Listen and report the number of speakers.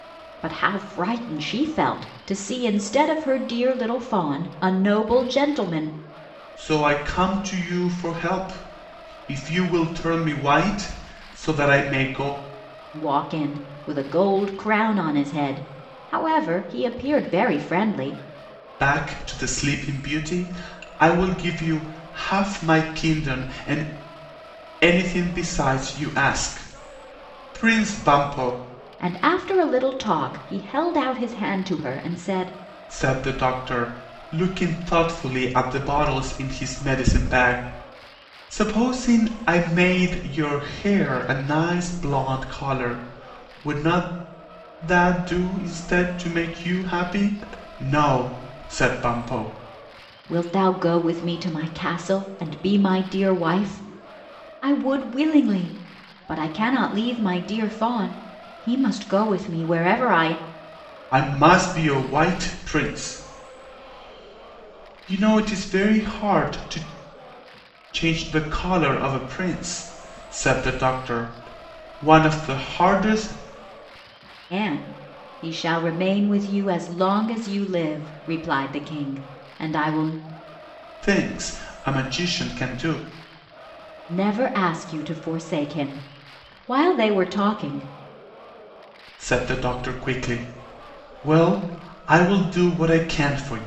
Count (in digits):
2